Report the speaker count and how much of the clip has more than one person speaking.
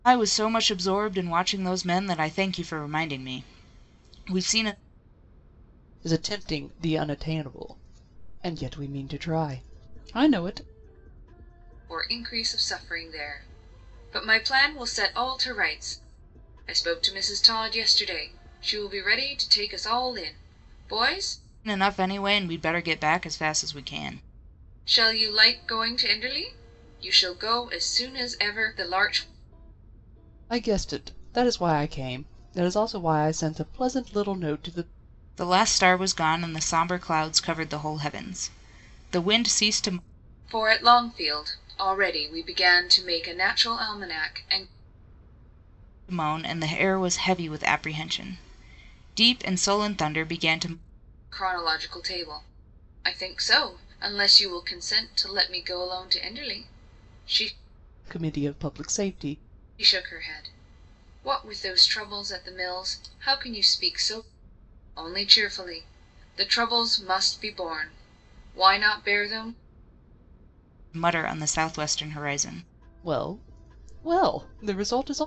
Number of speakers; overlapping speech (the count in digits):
3, no overlap